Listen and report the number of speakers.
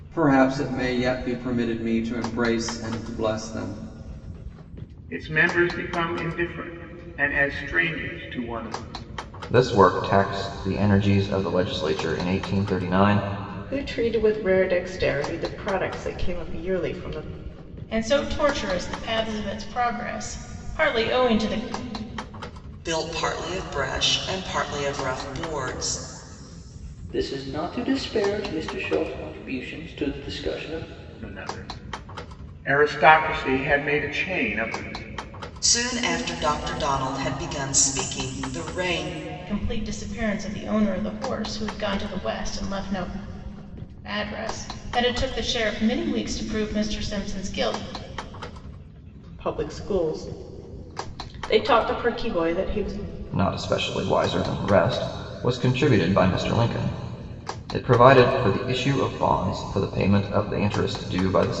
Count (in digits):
7